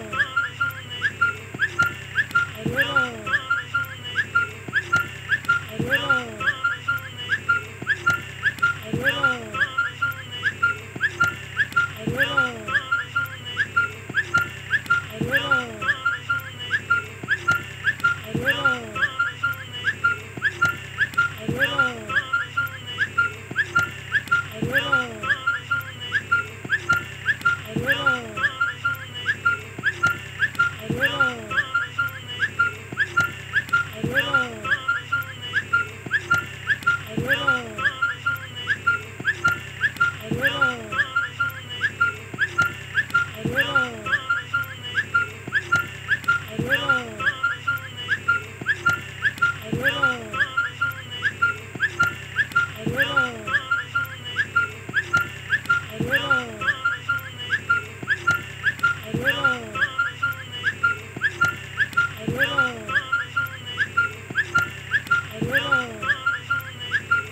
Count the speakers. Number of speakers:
0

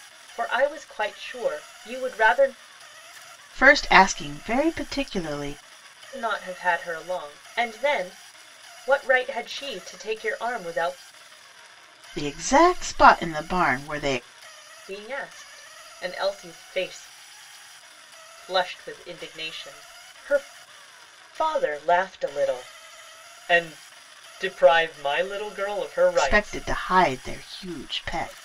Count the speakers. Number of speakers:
2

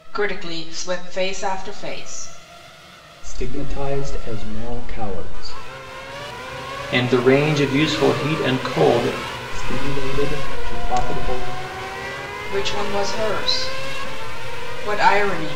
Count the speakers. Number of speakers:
3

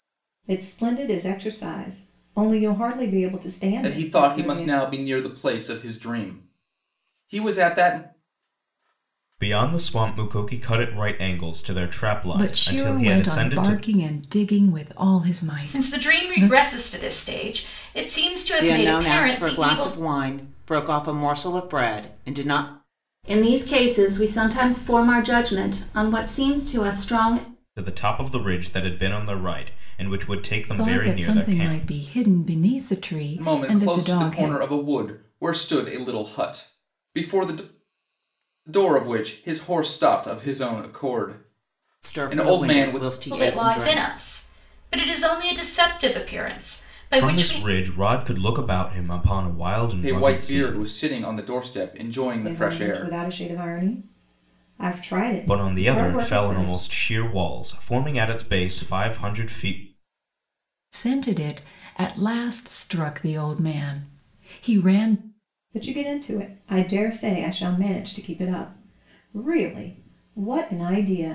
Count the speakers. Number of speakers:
7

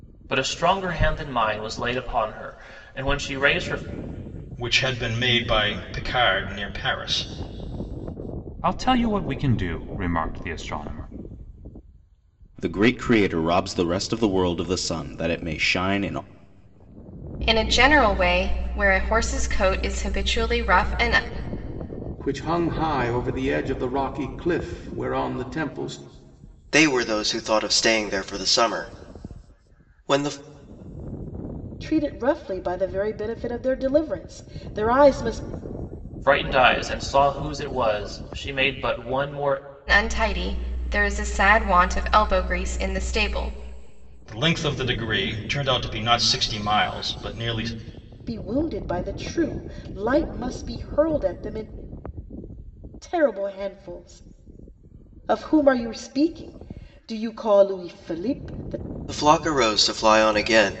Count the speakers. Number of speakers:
8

